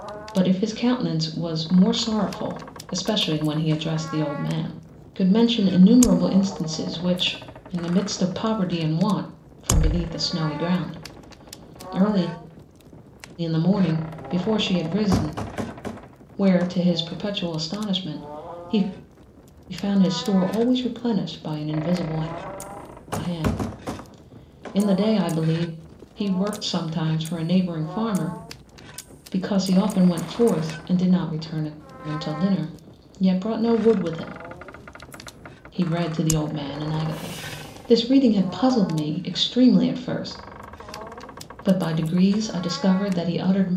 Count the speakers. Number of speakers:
1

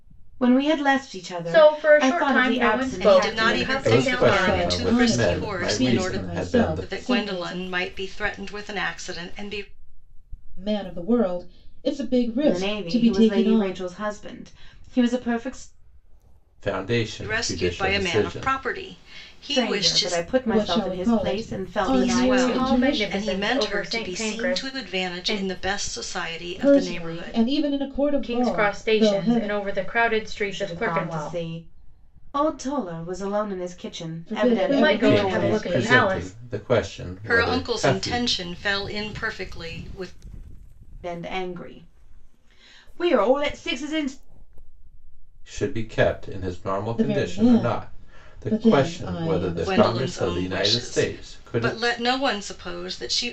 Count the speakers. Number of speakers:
5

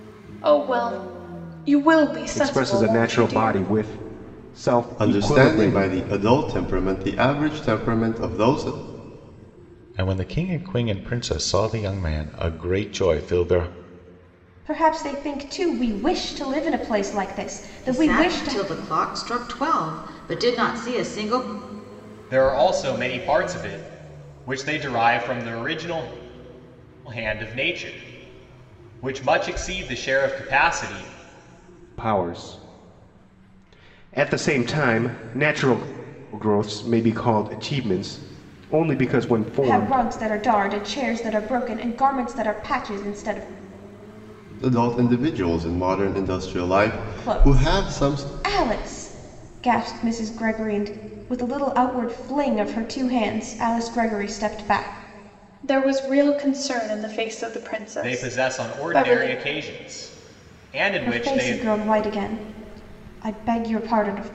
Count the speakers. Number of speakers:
7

